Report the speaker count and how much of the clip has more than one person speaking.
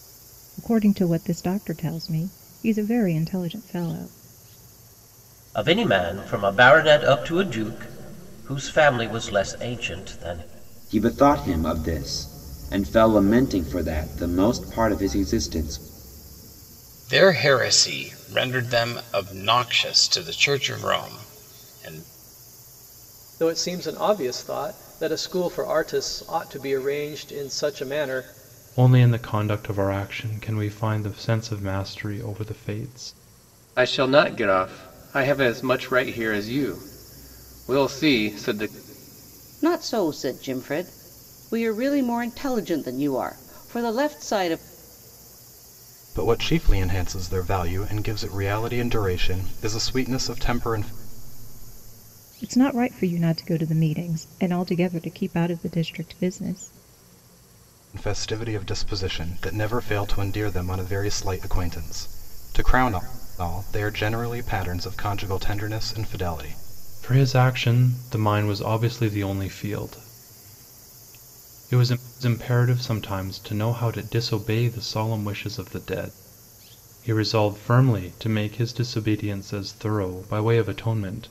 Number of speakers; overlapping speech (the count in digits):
9, no overlap